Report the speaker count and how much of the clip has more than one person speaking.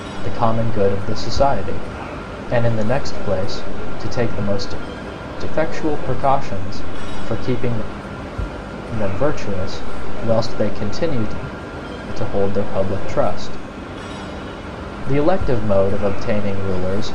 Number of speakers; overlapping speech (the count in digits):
1, no overlap